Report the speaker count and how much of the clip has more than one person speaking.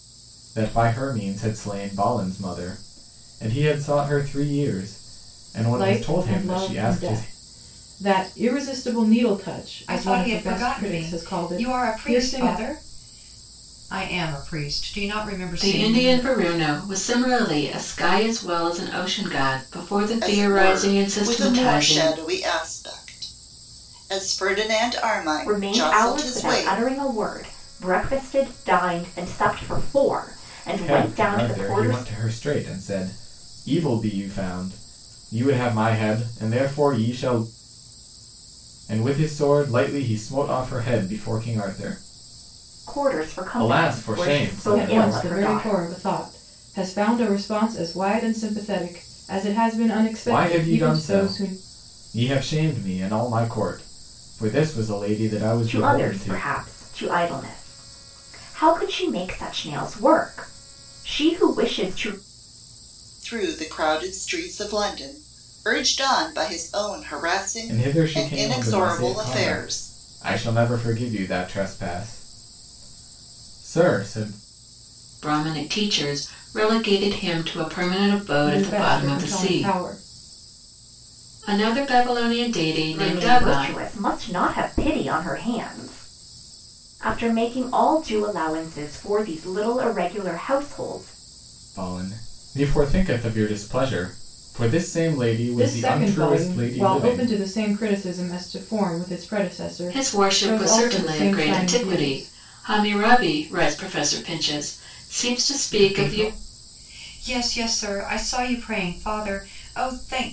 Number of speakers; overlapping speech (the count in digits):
6, about 22%